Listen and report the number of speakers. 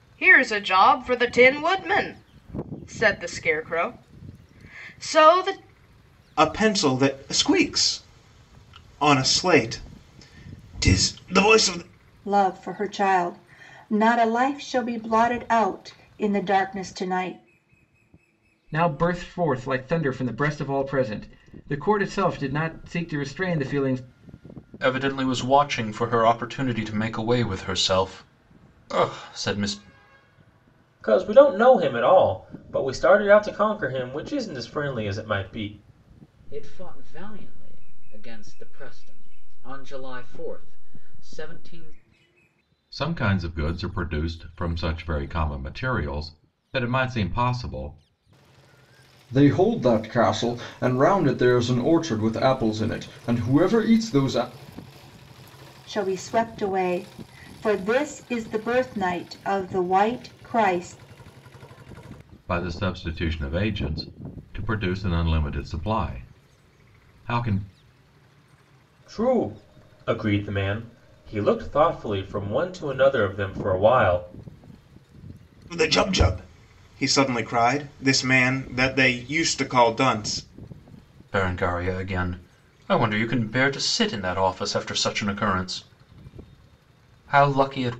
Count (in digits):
9